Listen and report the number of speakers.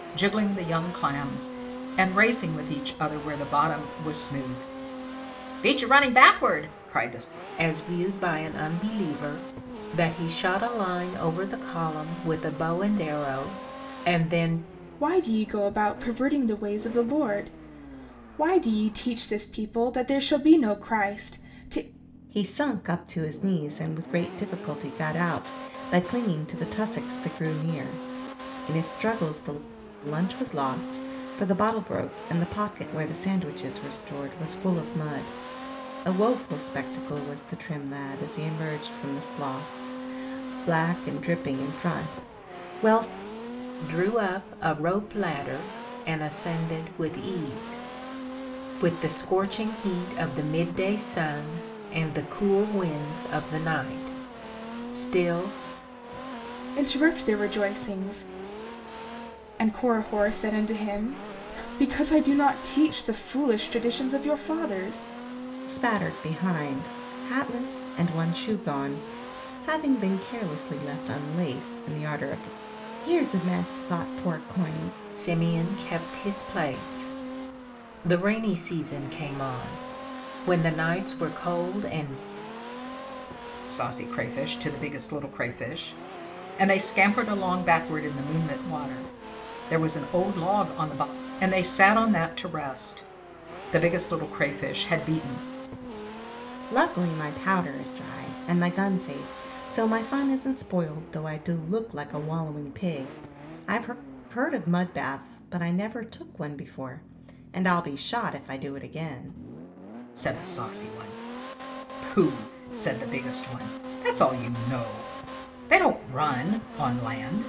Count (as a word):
four